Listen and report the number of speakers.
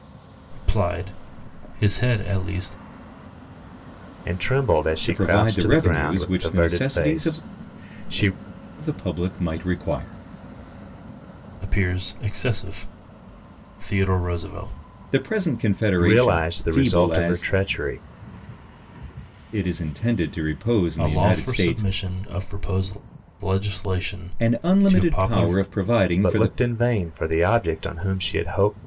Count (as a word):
three